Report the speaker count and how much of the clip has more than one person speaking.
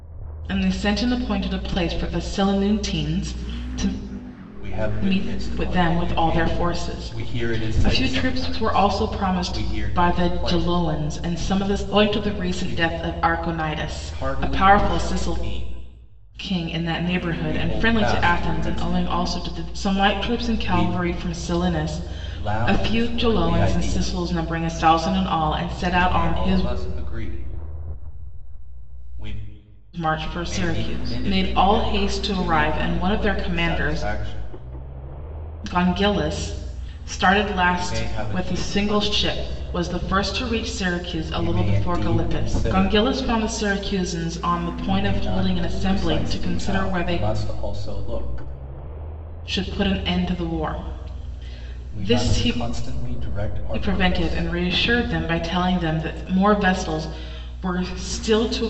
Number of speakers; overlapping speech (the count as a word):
two, about 43%